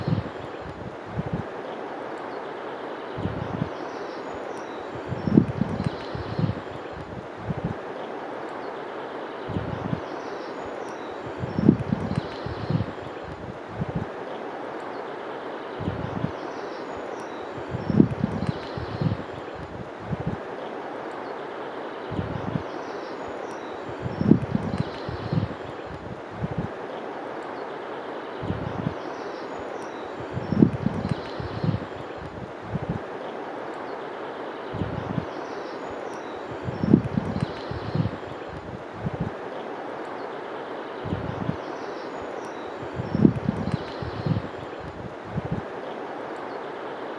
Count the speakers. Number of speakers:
zero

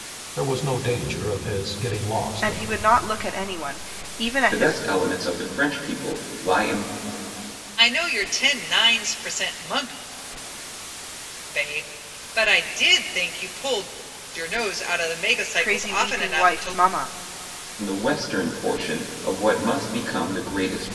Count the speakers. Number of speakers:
four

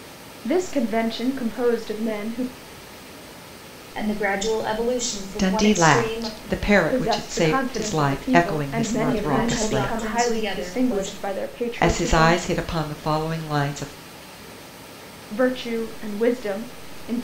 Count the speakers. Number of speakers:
three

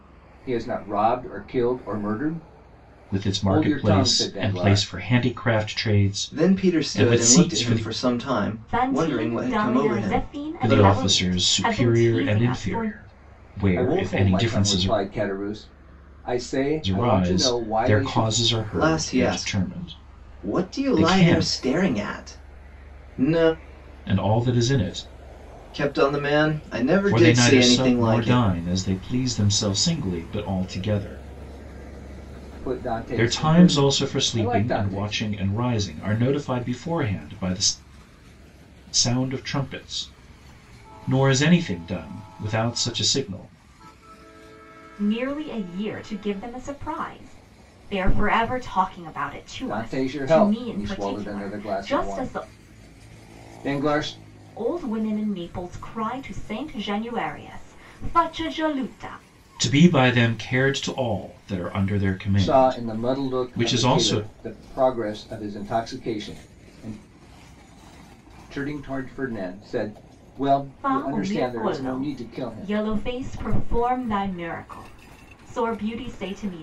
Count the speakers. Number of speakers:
four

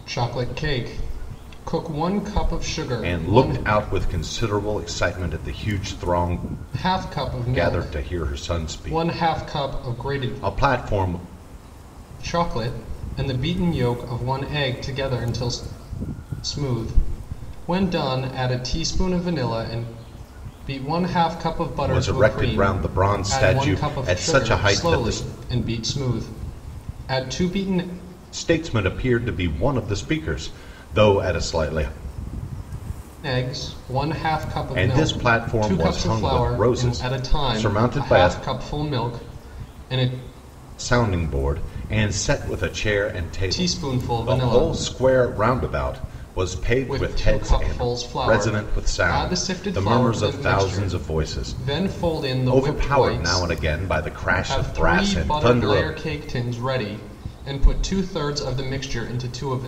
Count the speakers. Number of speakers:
two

